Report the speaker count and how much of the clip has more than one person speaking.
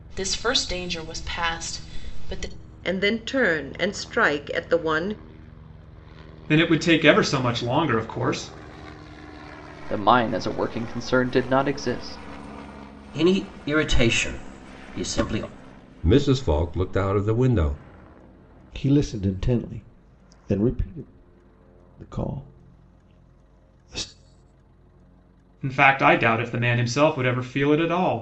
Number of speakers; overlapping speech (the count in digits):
7, no overlap